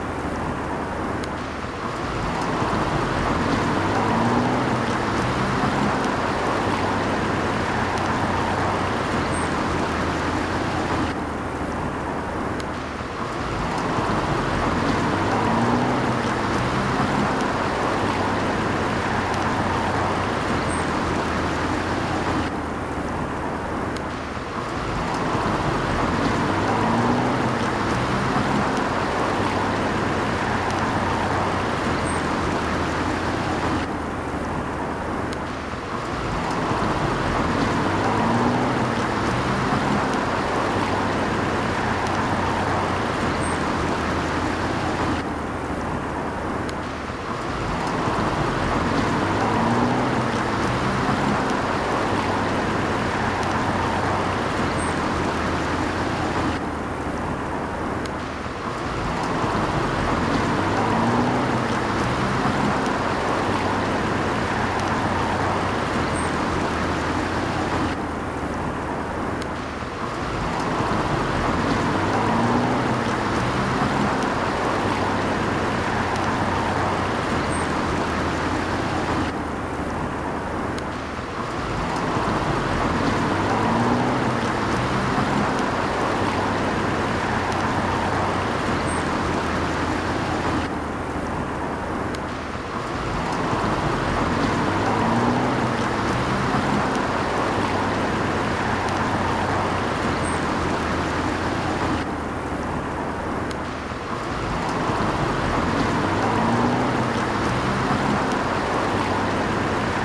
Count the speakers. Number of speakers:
0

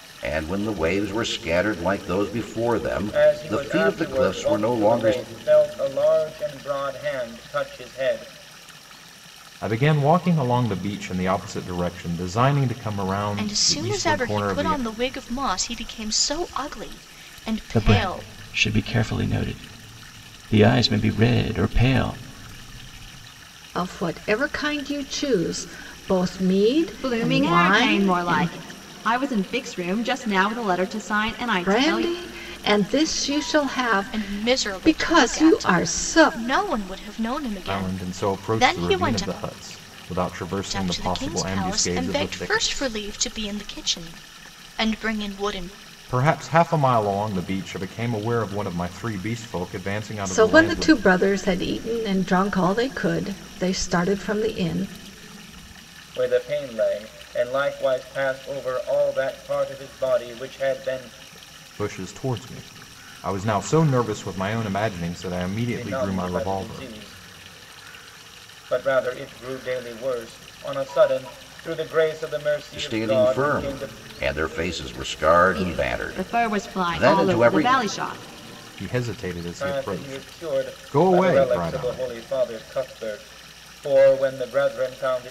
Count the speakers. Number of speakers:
7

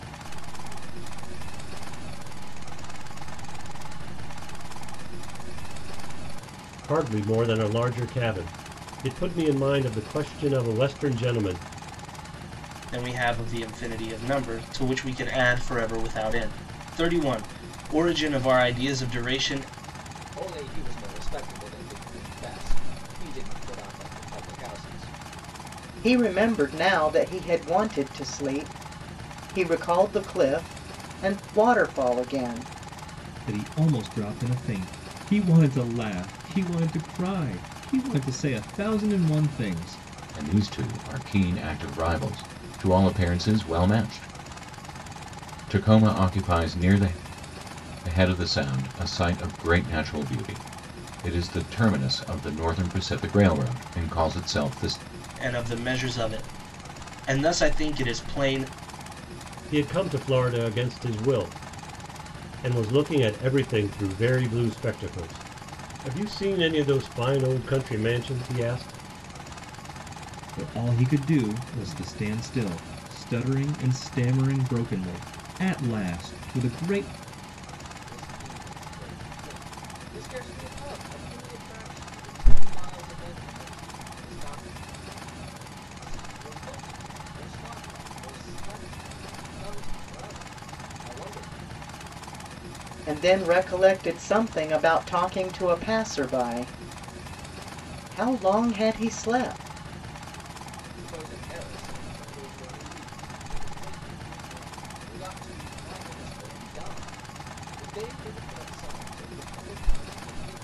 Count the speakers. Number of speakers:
7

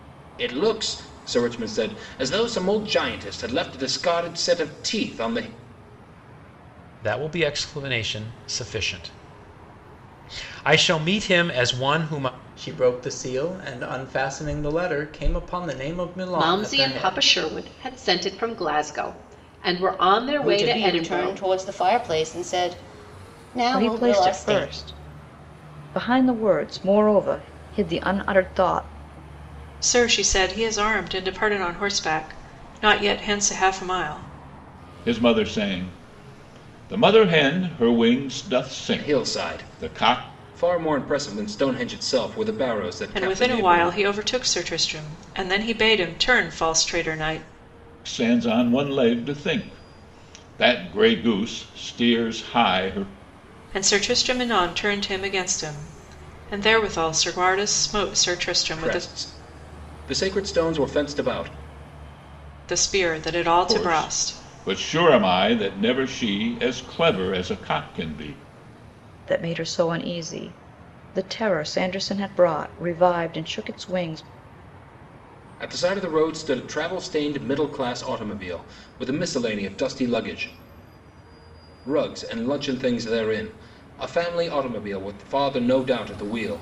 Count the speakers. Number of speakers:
8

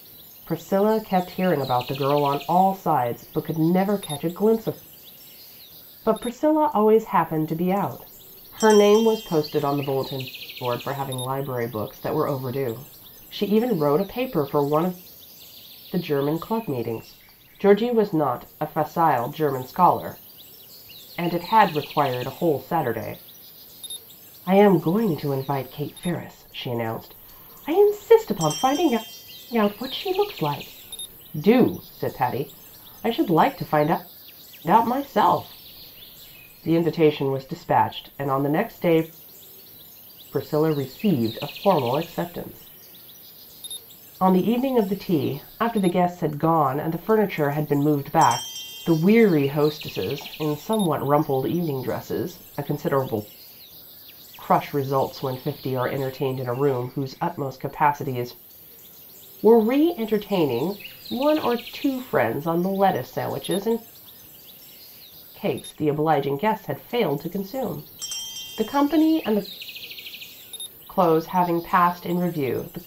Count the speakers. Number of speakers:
1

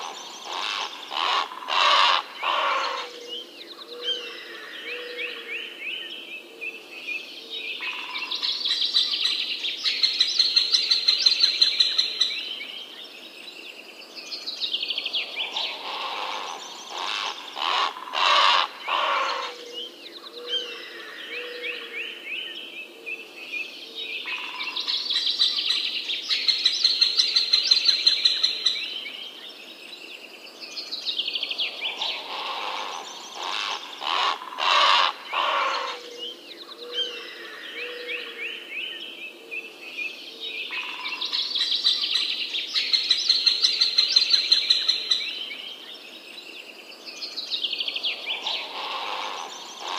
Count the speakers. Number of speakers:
0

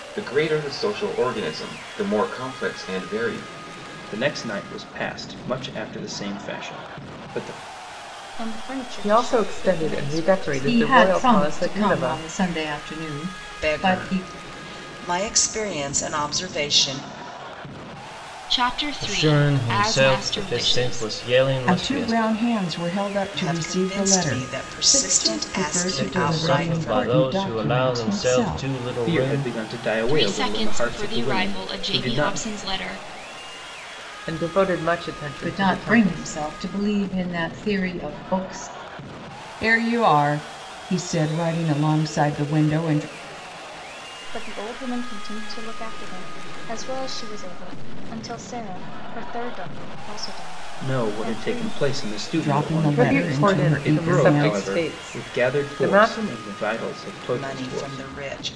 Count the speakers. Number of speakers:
9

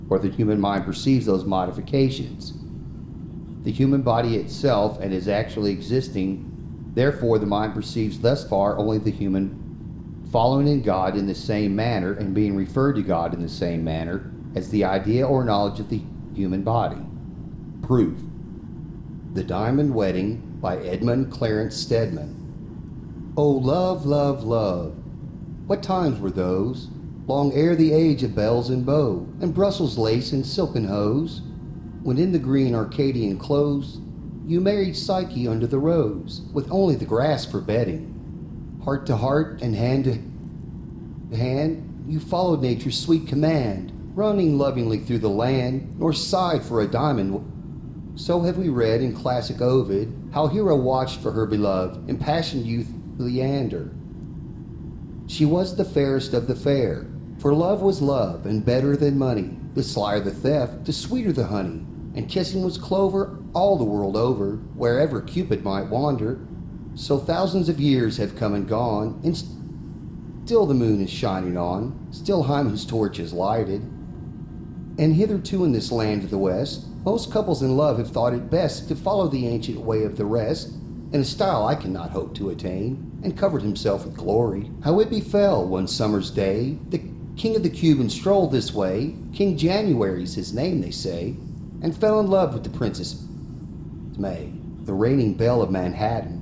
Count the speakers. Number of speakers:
1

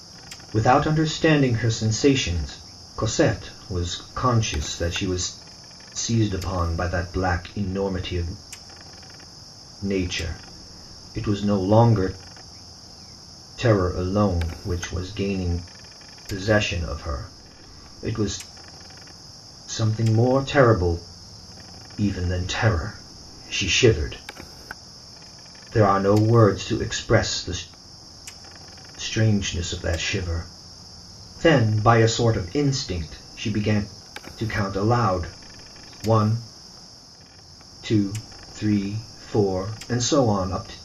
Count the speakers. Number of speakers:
1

